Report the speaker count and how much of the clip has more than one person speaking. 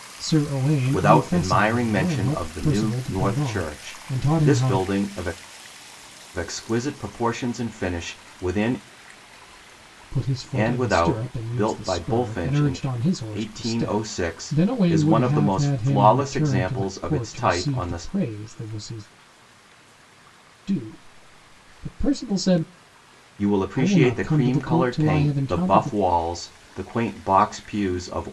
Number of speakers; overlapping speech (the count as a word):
two, about 46%